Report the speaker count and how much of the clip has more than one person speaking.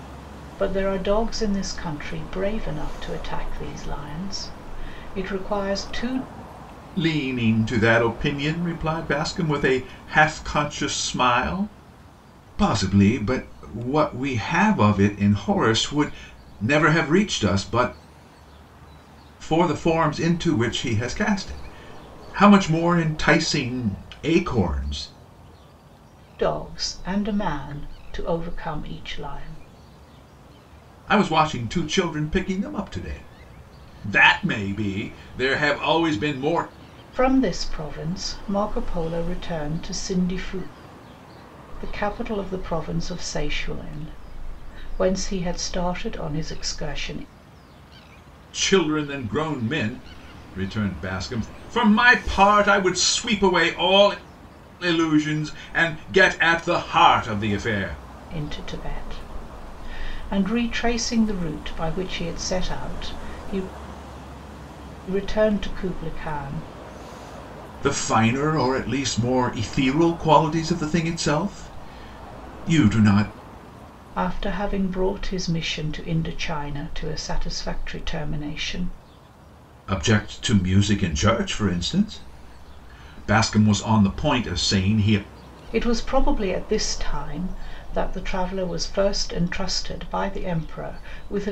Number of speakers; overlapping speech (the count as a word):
two, no overlap